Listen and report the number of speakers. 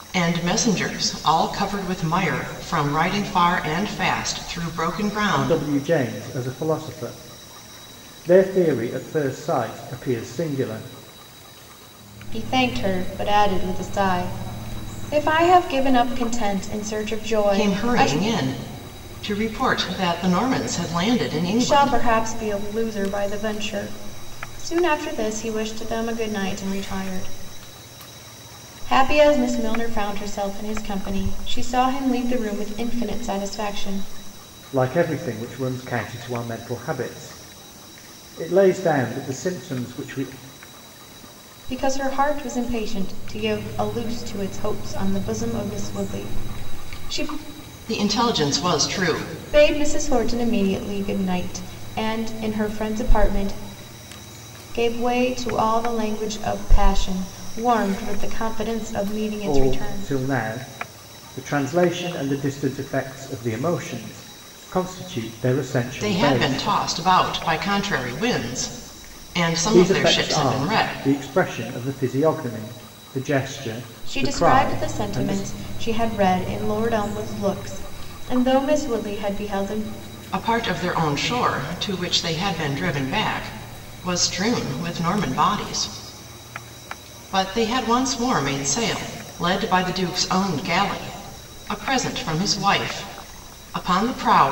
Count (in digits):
3